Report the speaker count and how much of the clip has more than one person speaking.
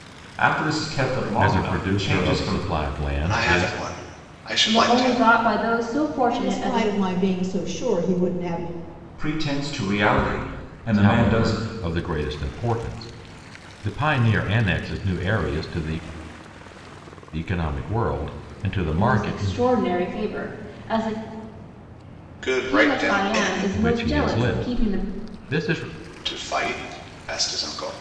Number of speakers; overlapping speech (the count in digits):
5, about 25%